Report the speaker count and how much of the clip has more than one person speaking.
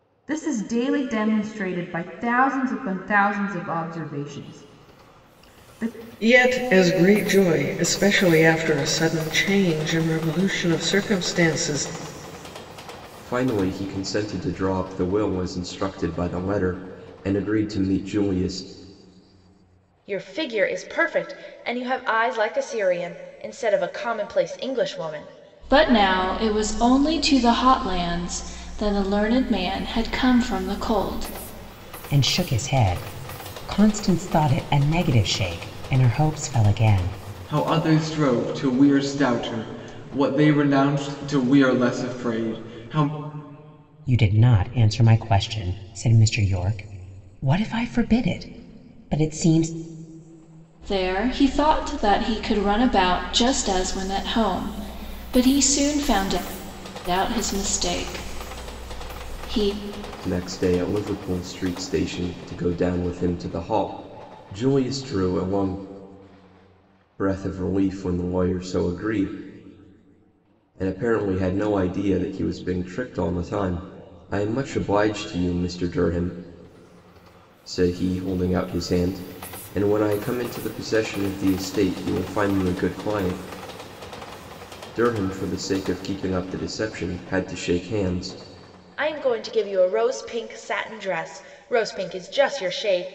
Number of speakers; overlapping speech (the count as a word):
seven, no overlap